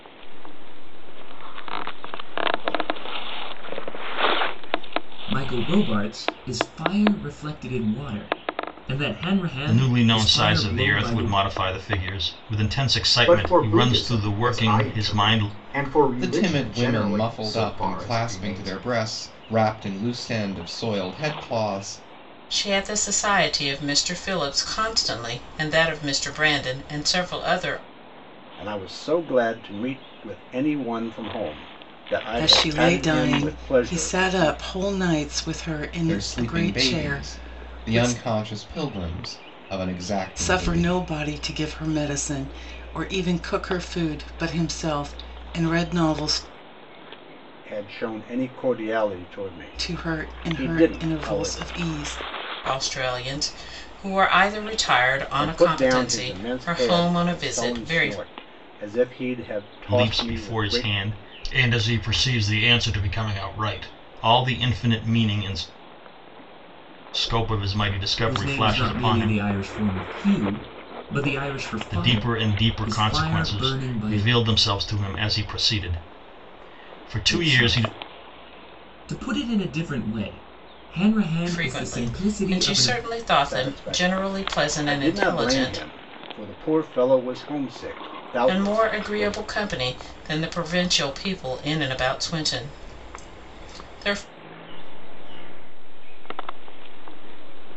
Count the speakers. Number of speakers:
8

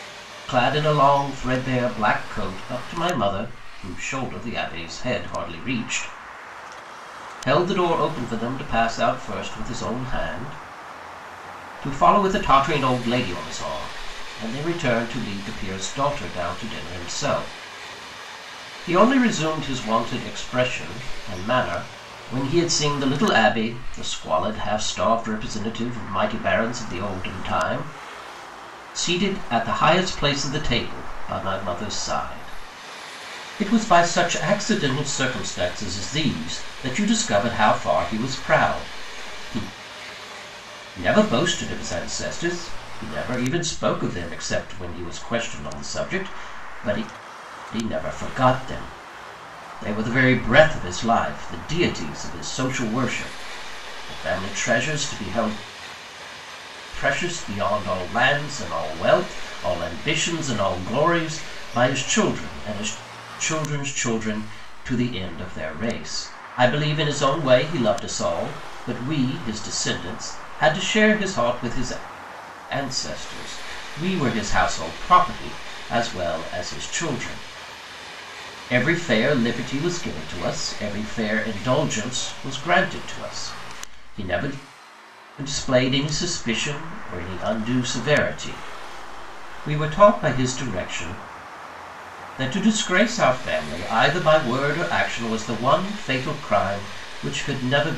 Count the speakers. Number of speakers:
1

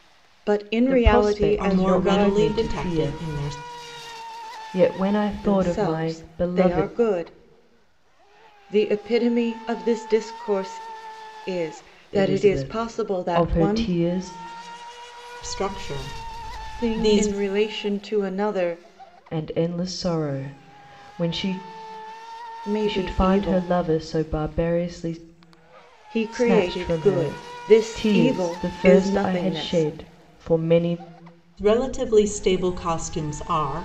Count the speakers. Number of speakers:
3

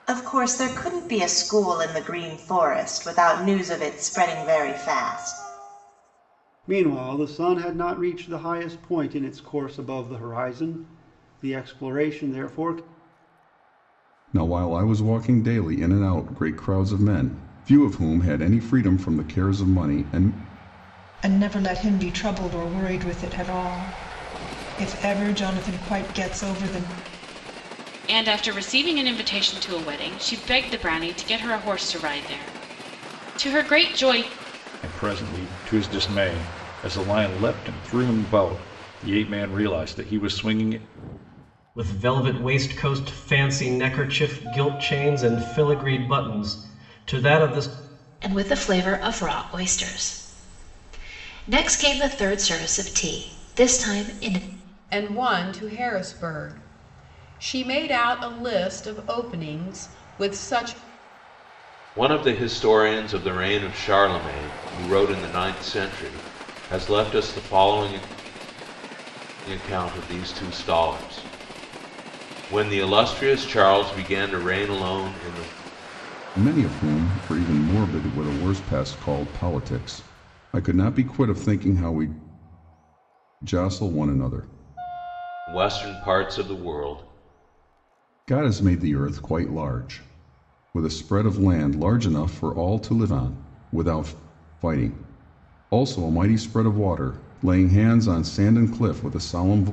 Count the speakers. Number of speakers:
10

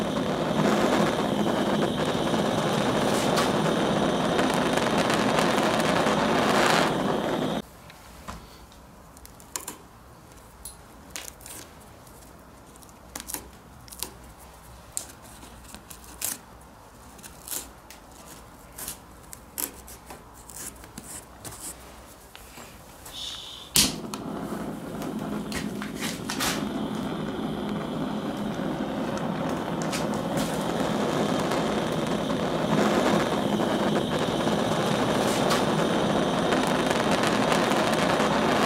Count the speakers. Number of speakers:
0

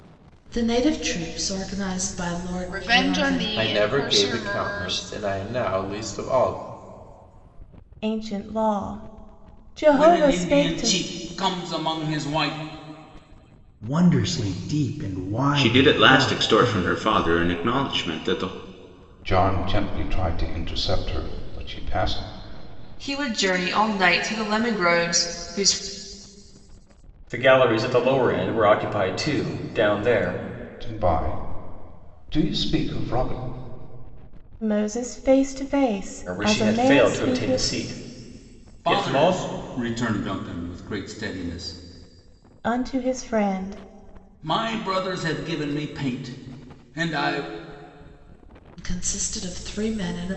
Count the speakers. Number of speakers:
10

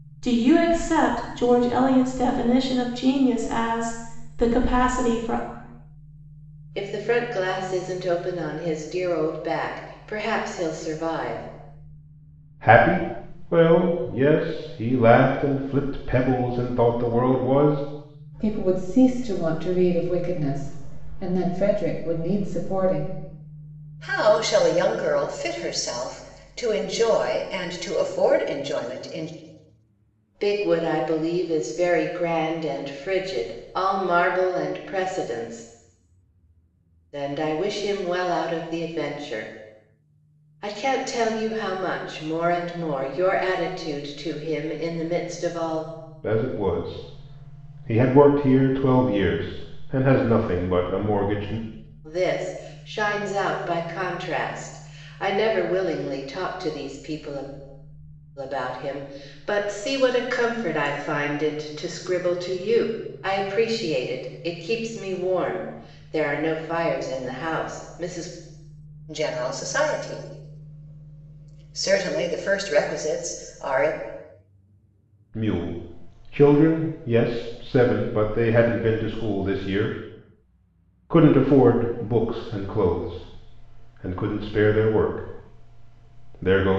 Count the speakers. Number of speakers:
5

